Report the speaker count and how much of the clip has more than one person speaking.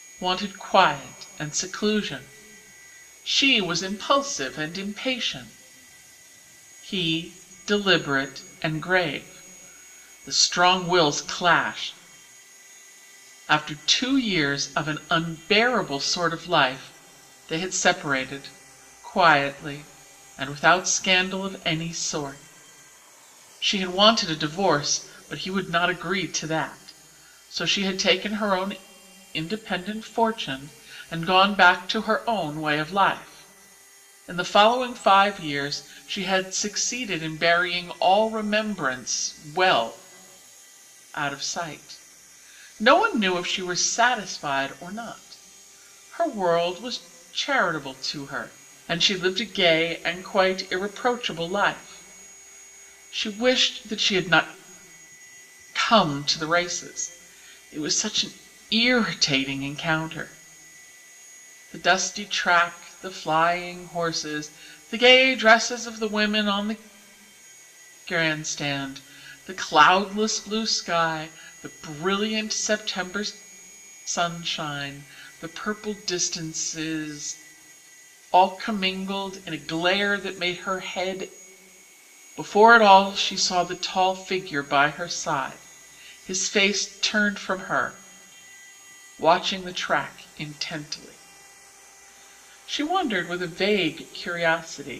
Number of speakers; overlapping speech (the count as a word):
one, no overlap